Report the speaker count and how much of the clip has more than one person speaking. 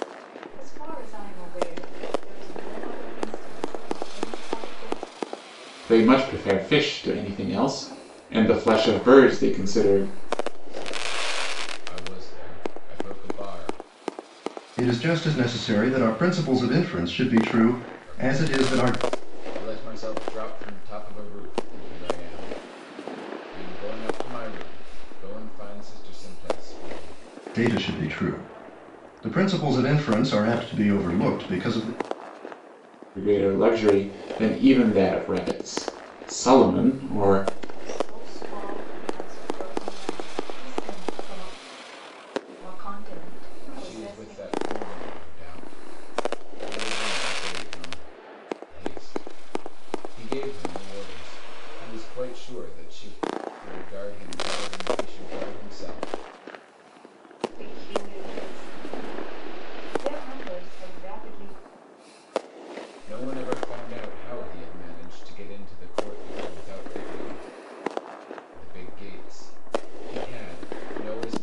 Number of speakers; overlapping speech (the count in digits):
4, about 4%